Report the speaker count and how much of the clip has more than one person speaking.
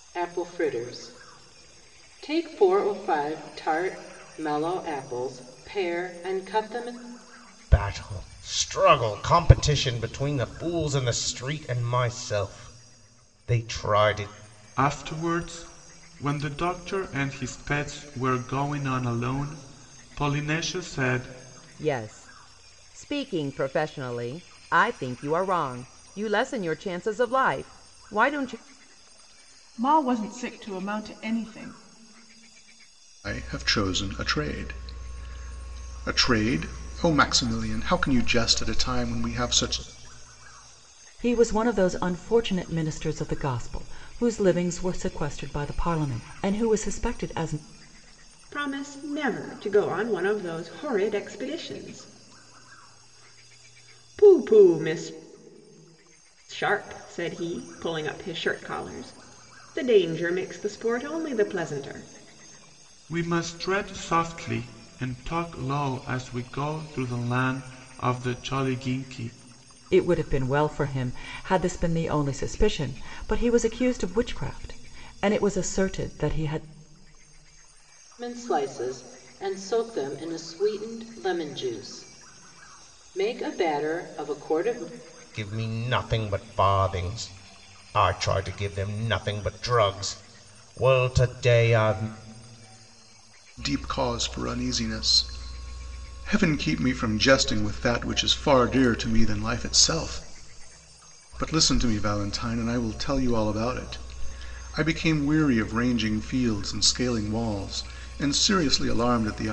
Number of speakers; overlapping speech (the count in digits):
8, no overlap